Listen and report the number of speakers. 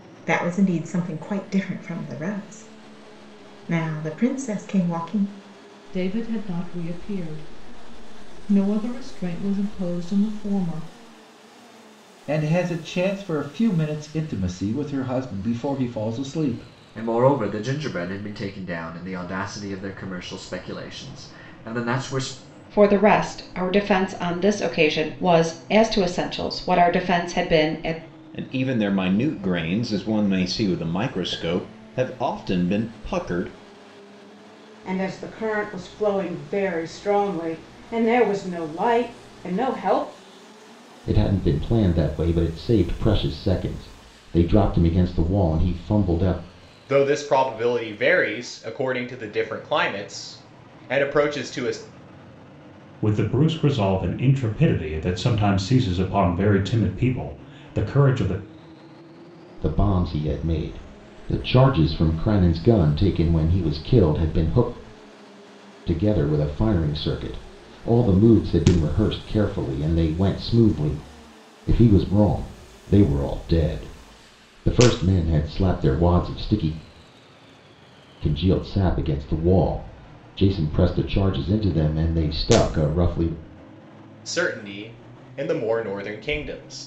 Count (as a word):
ten